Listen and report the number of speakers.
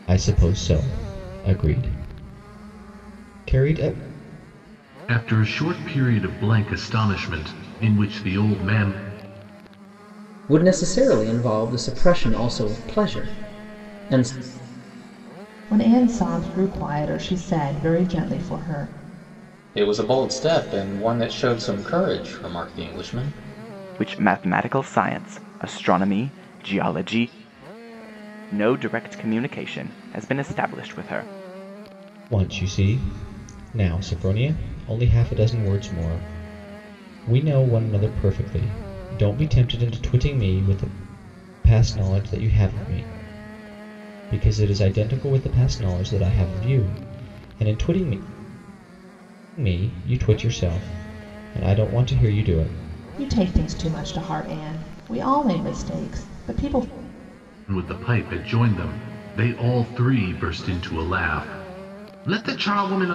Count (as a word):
six